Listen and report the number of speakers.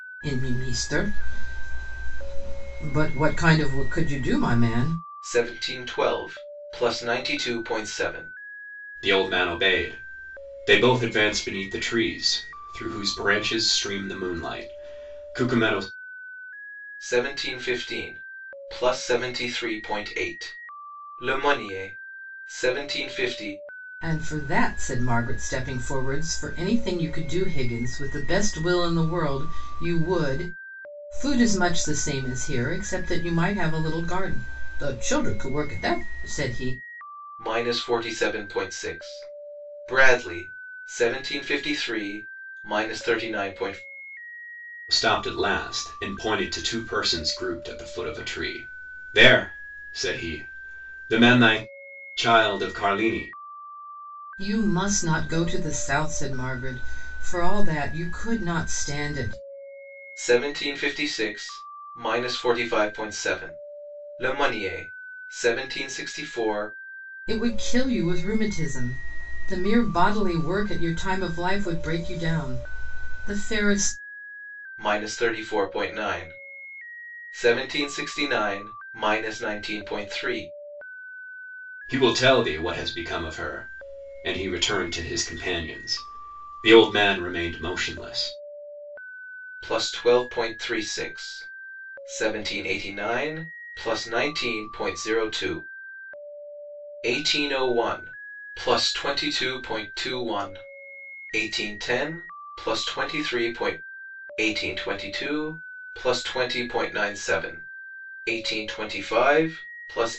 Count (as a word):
three